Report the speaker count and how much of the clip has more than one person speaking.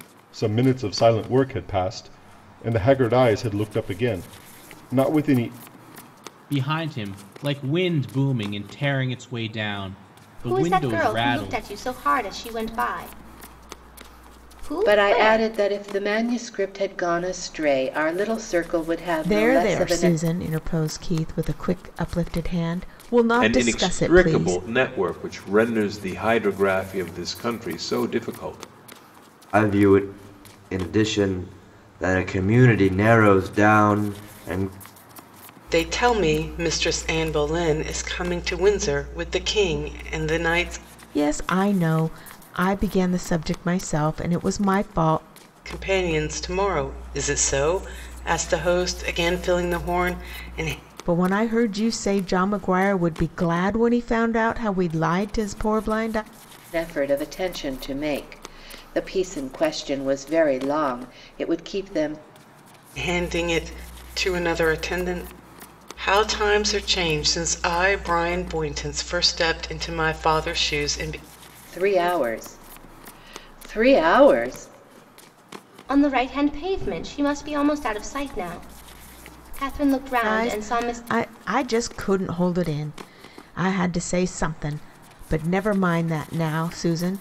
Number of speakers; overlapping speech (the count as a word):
eight, about 6%